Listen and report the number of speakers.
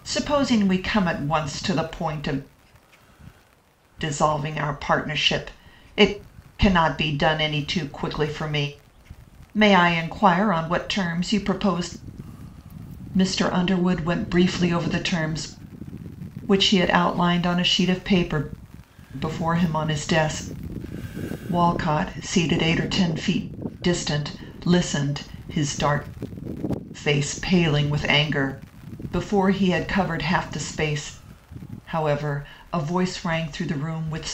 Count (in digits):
1